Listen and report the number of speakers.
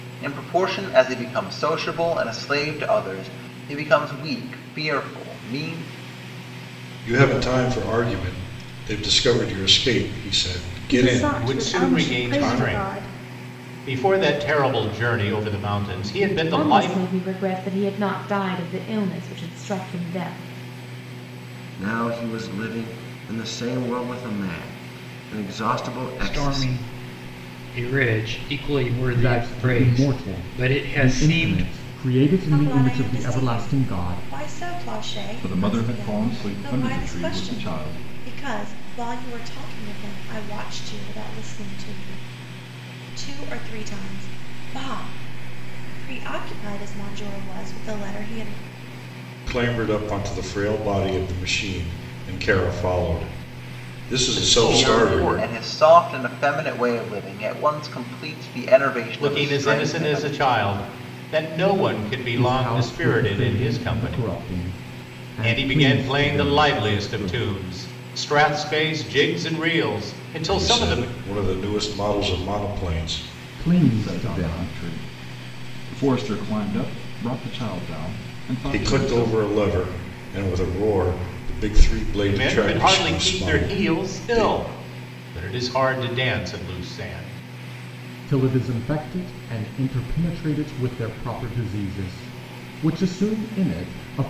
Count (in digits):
10